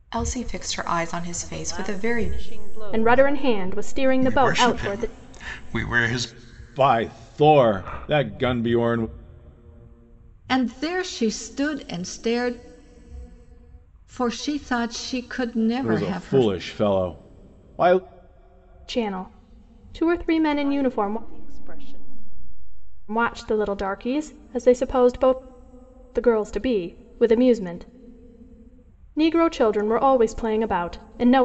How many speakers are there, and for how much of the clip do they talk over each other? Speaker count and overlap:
6, about 13%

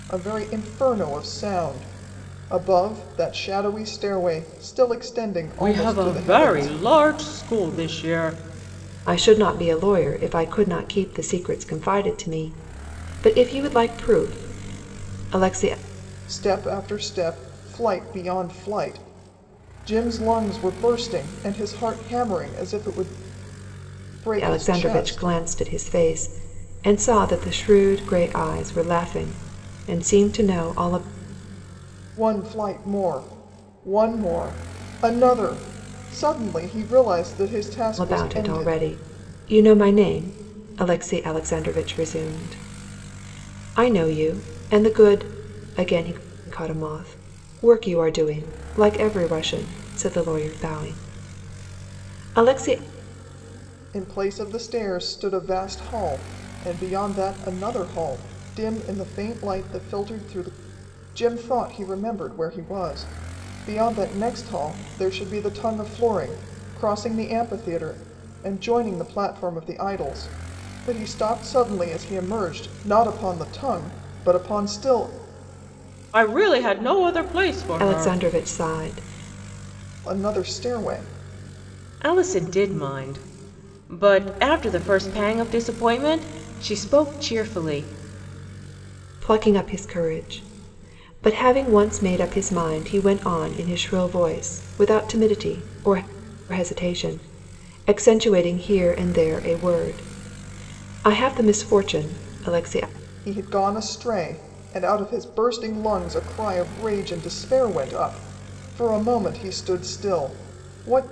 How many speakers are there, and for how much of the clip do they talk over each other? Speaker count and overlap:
3, about 3%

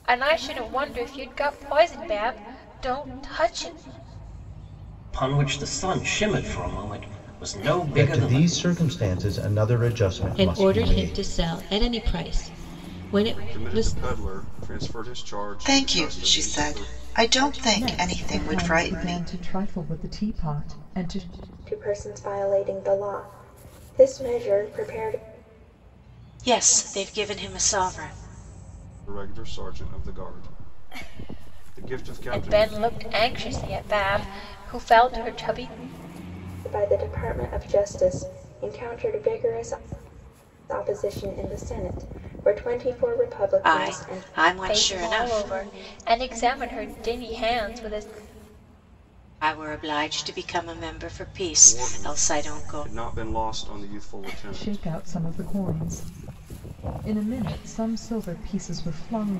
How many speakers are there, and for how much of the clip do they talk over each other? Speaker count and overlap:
9, about 14%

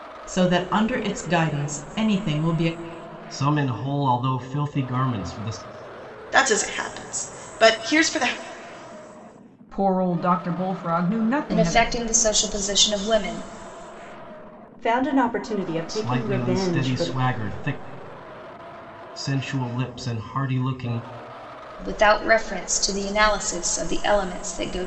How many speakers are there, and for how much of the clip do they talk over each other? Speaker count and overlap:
6, about 7%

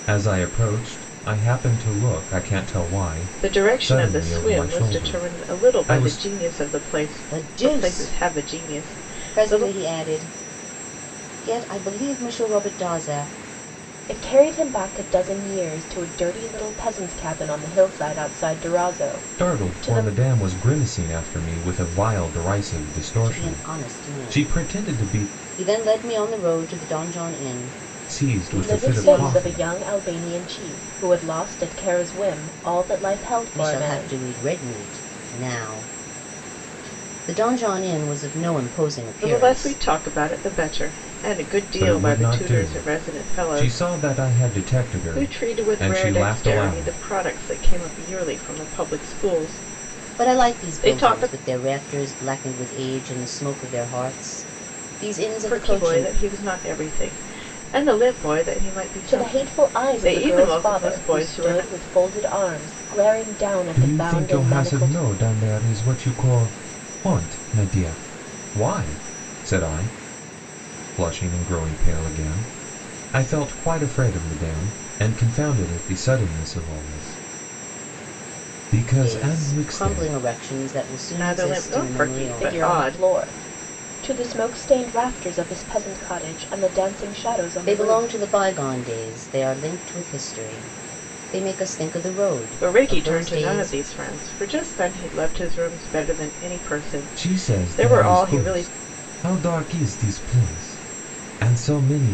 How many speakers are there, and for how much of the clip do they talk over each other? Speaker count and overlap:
4, about 27%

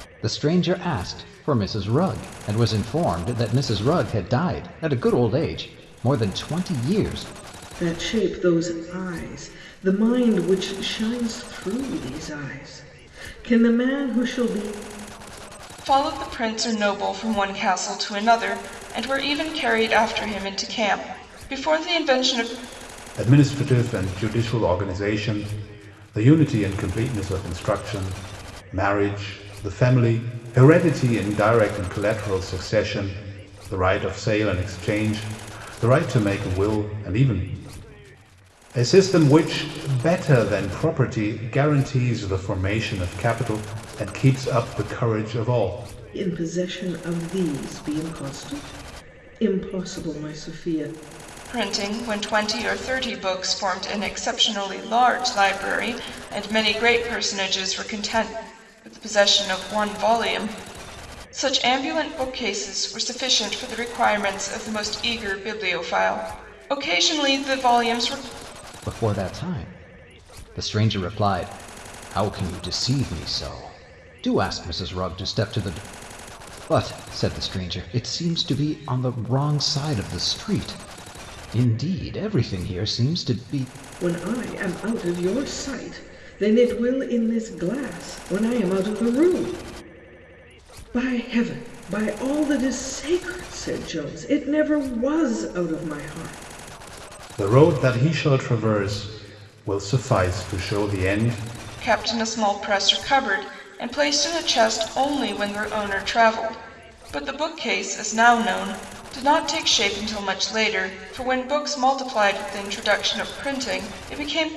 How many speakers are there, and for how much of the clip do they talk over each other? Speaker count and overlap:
4, no overlap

